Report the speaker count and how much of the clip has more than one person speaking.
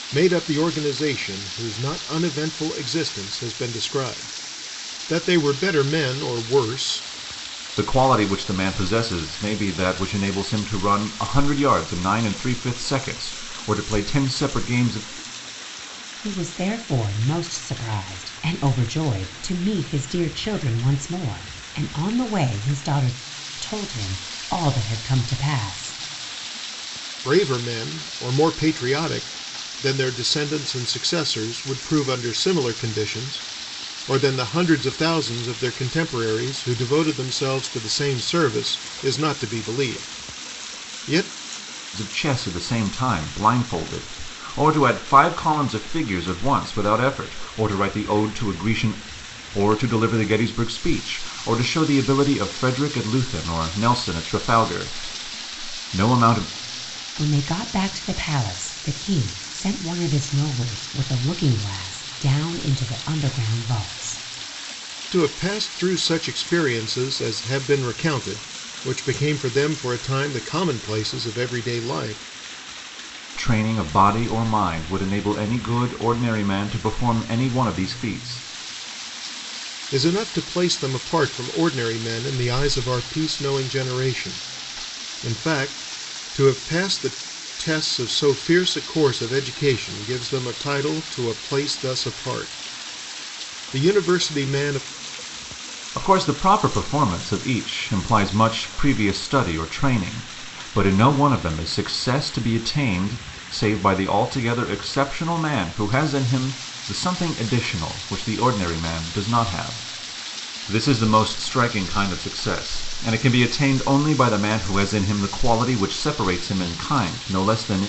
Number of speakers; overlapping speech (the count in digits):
3, no overlap